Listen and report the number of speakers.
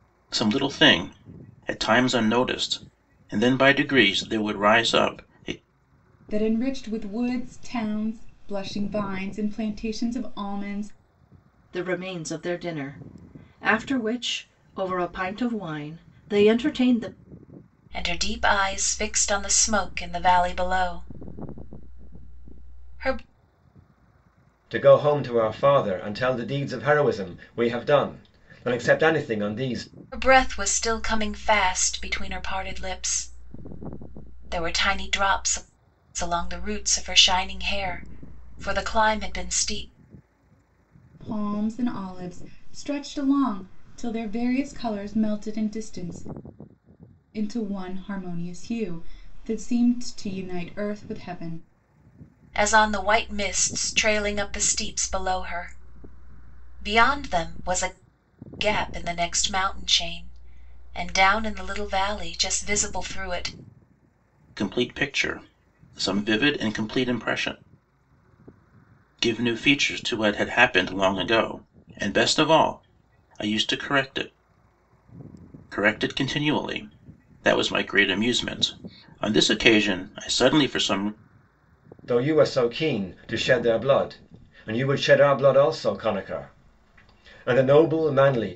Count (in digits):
5